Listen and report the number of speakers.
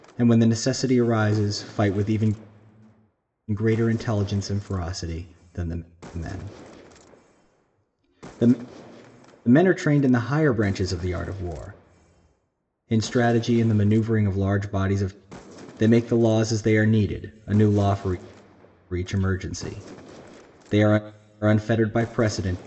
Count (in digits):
1